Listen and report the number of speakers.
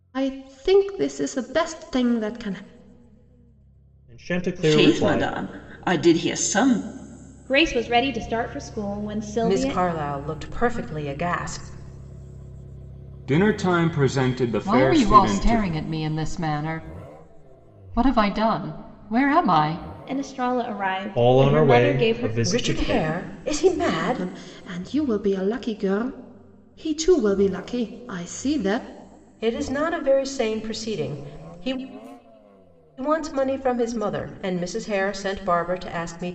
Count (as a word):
seven